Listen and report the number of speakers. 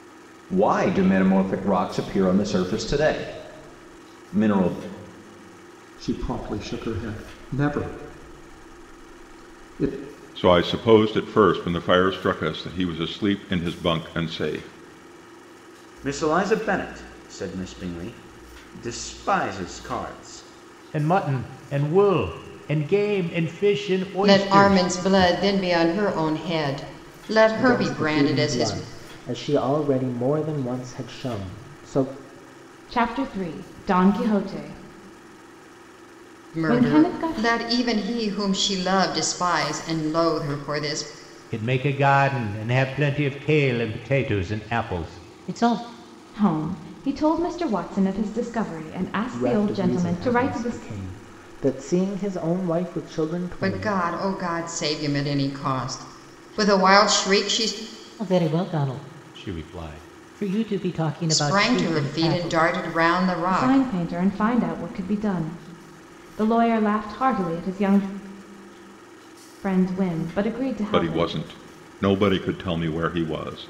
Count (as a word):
eight